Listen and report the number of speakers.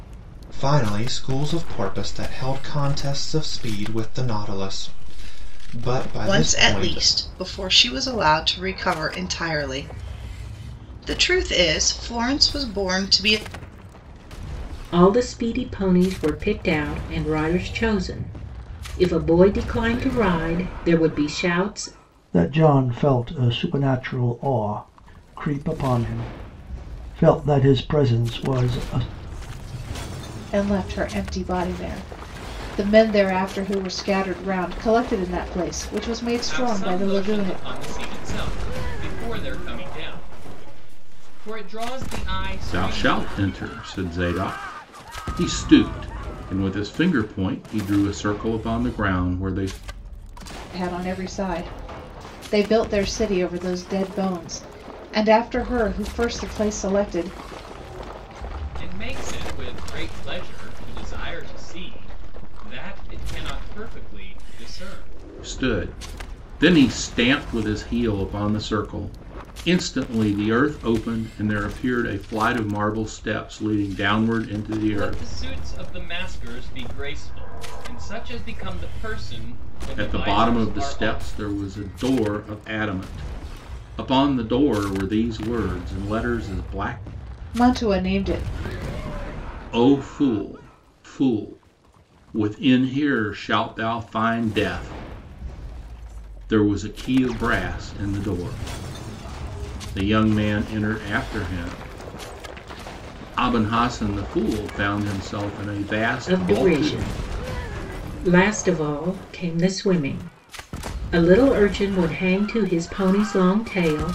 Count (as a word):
seven